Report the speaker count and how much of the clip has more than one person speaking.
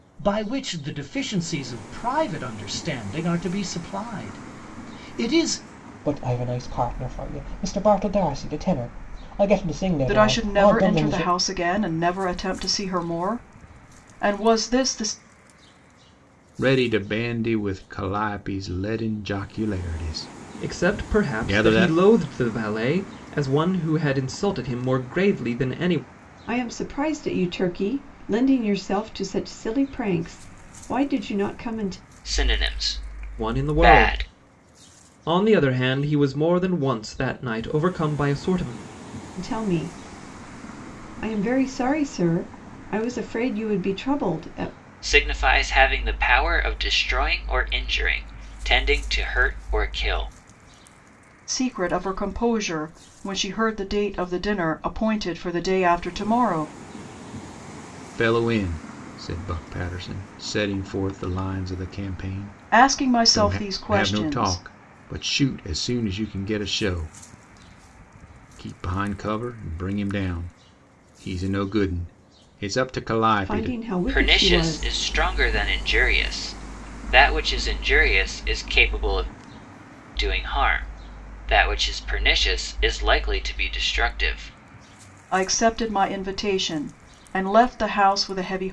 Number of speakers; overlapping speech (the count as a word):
seven, about 7%